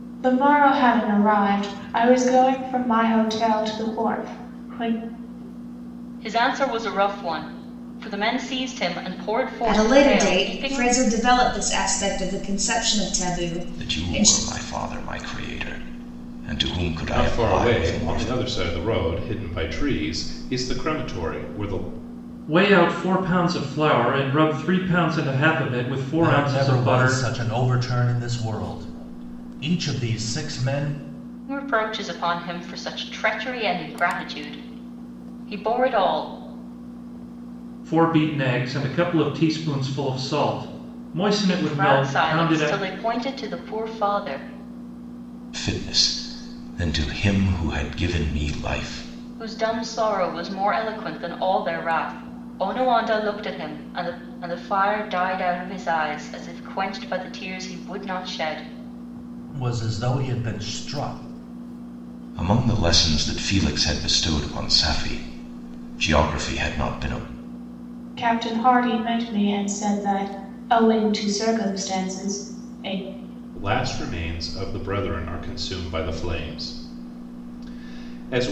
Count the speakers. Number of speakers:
7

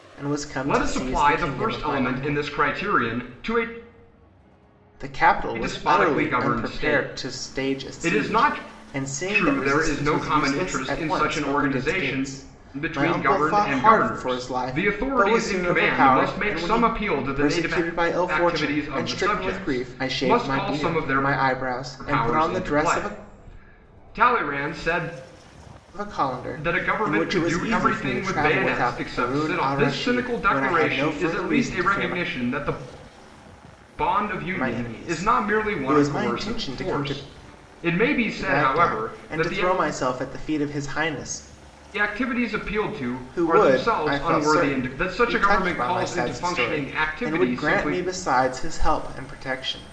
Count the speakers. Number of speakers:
2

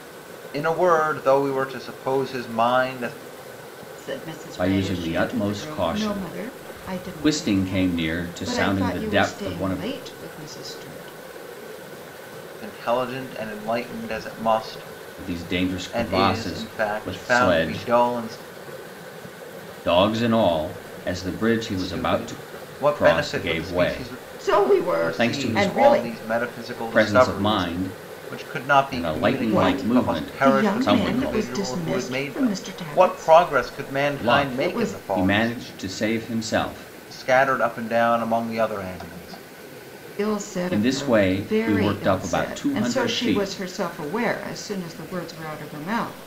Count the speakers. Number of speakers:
3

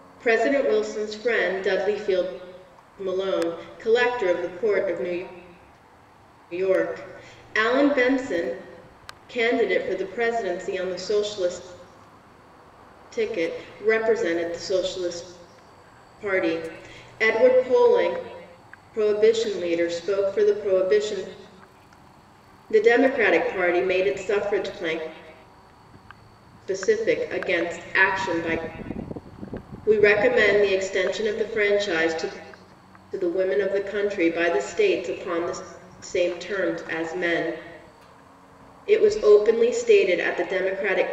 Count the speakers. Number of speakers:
1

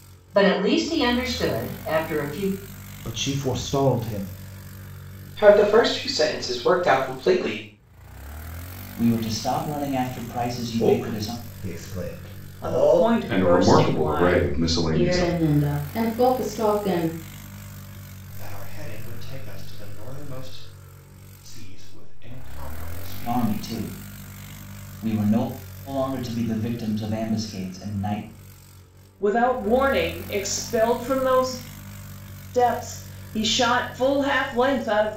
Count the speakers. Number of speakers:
9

